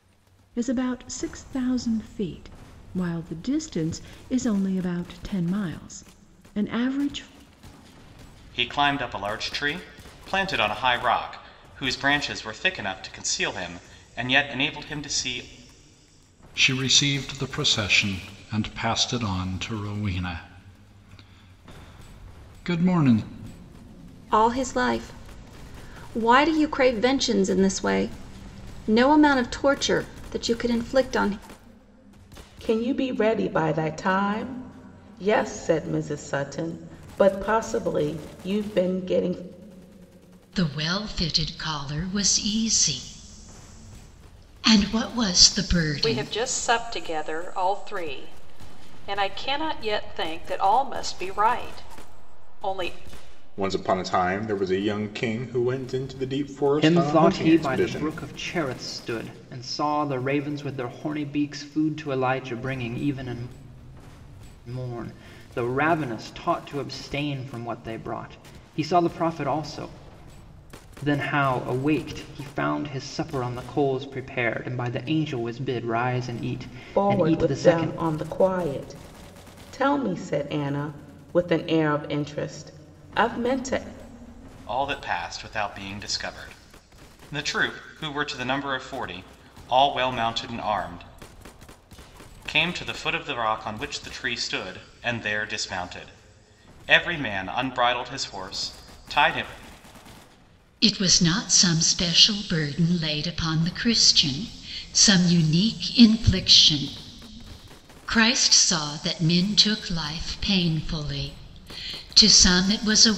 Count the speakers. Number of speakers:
nine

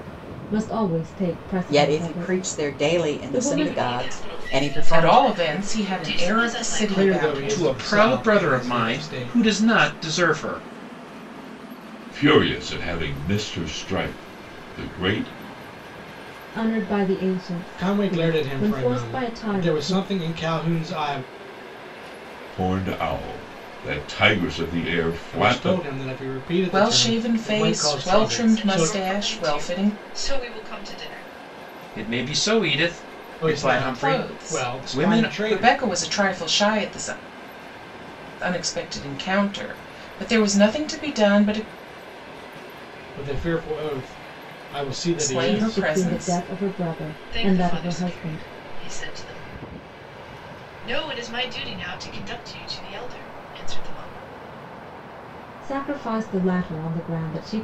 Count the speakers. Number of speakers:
seven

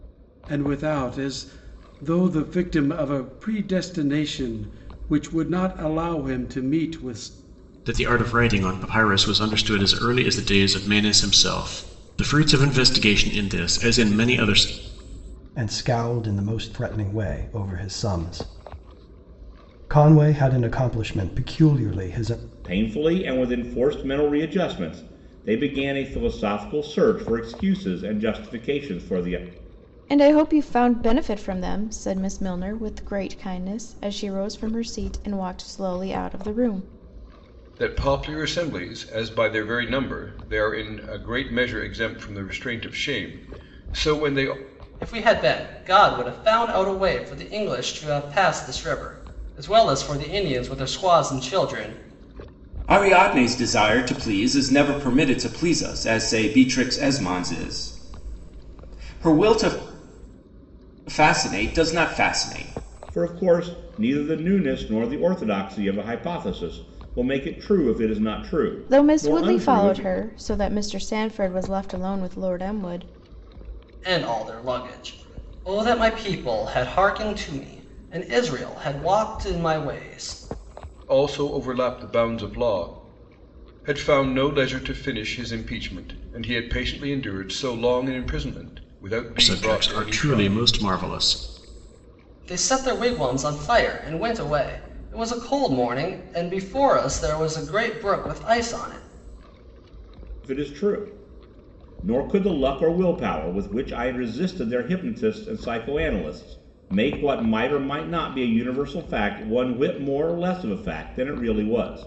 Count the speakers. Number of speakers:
eight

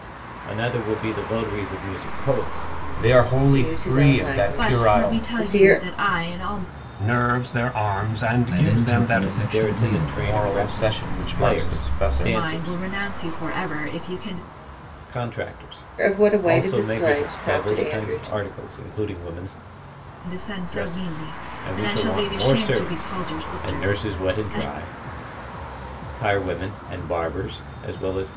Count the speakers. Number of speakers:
seven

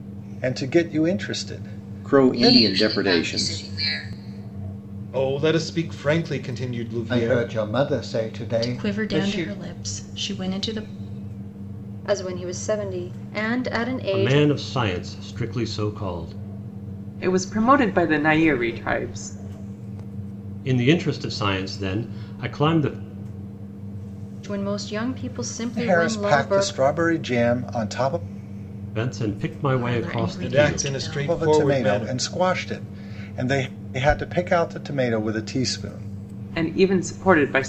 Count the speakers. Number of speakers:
nine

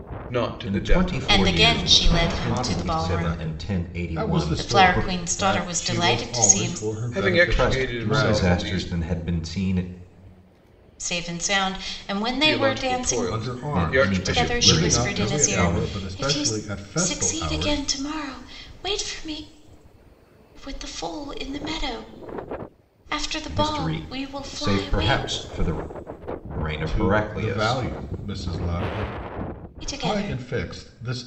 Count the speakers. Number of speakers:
four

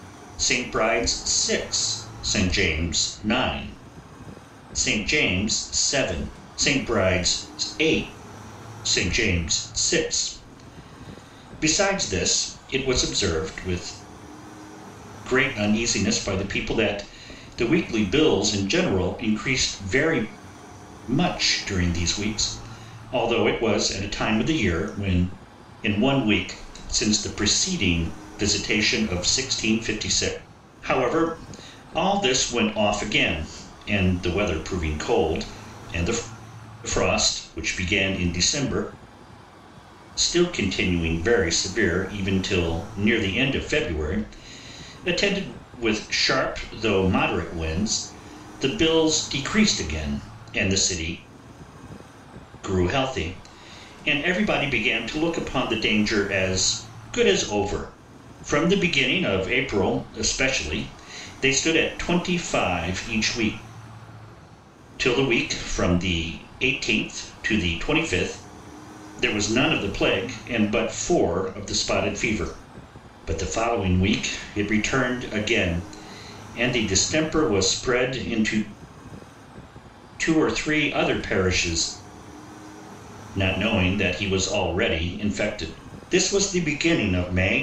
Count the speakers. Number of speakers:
one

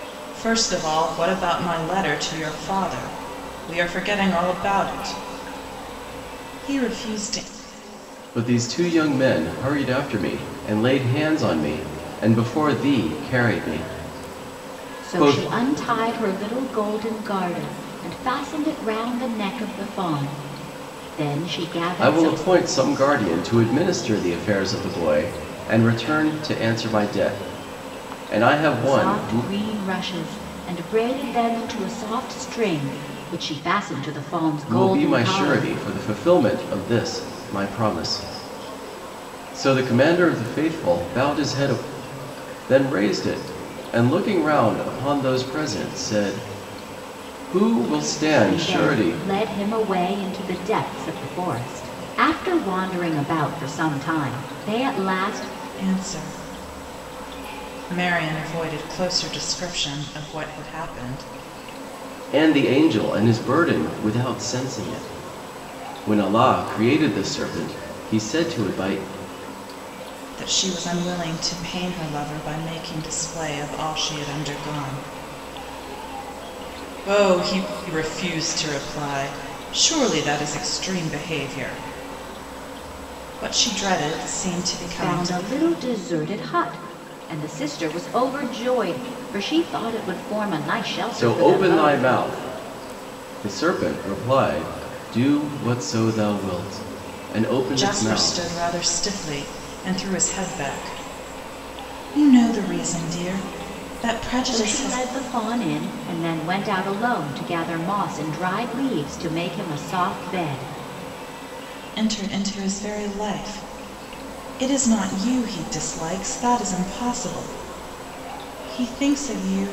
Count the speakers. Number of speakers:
three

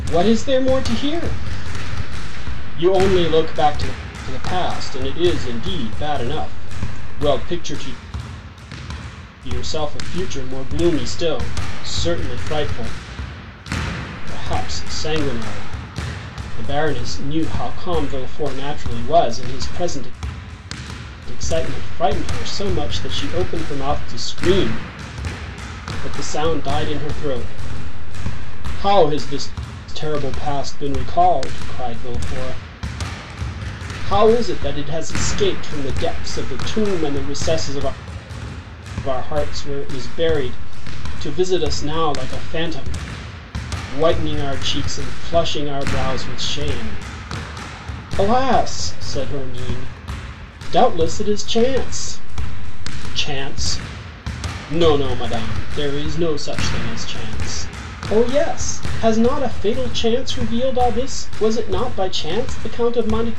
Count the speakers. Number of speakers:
one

